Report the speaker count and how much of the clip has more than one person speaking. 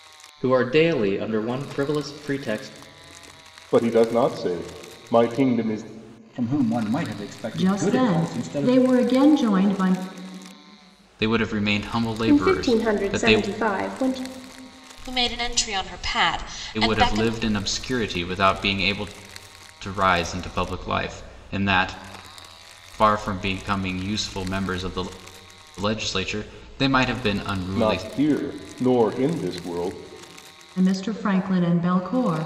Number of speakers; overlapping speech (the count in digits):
7, about 10%